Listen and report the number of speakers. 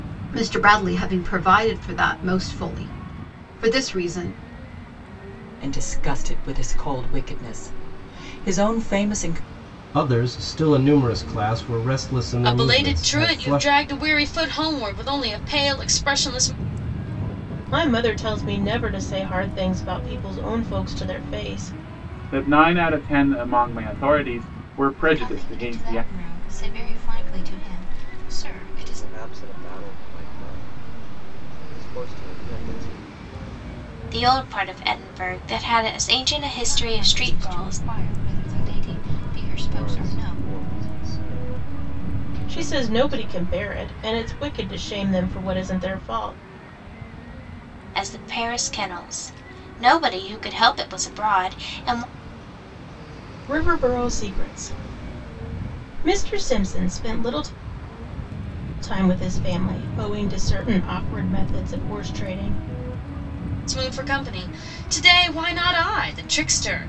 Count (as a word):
nine